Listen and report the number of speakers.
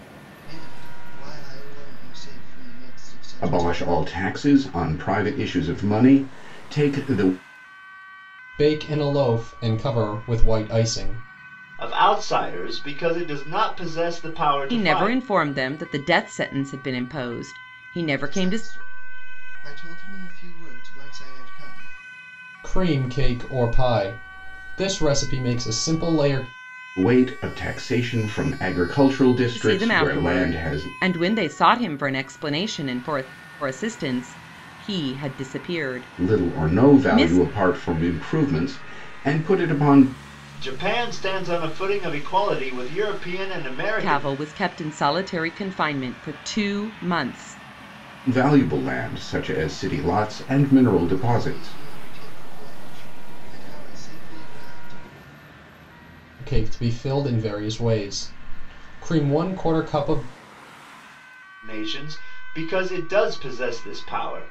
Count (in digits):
5